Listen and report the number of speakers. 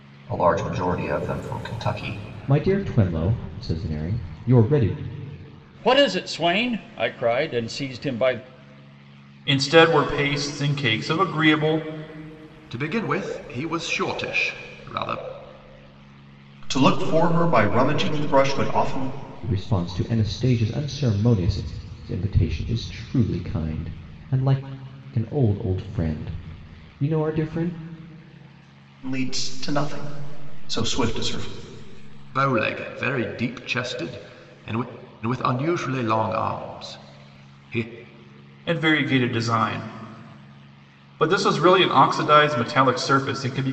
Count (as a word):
six